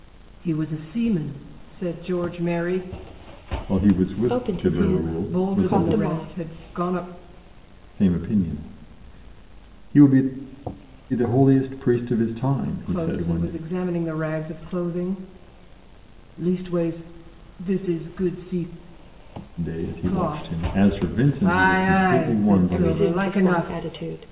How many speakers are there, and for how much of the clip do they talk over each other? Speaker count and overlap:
3, about 28%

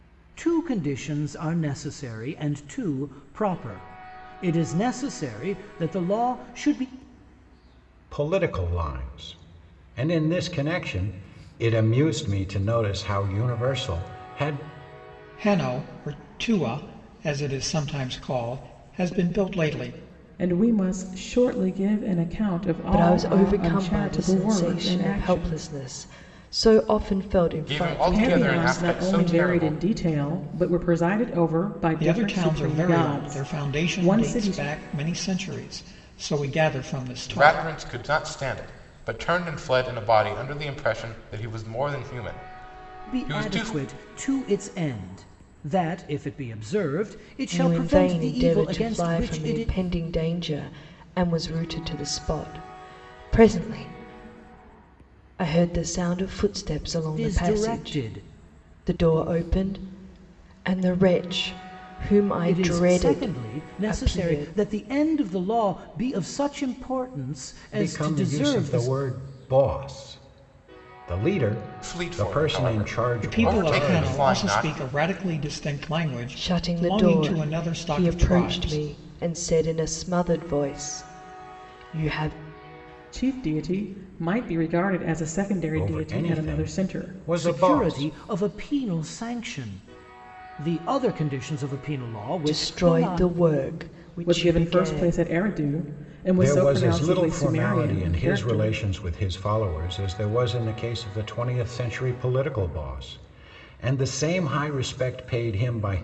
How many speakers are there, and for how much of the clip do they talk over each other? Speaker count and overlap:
6, about 26%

